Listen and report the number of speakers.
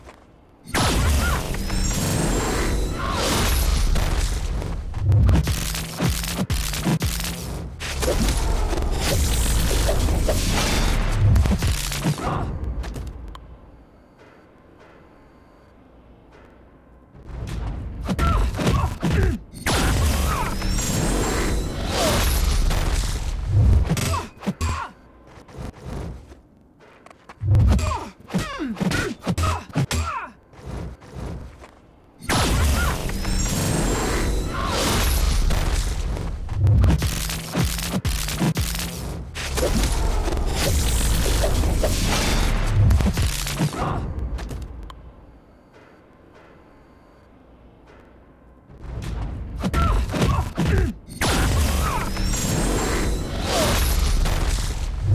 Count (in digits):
0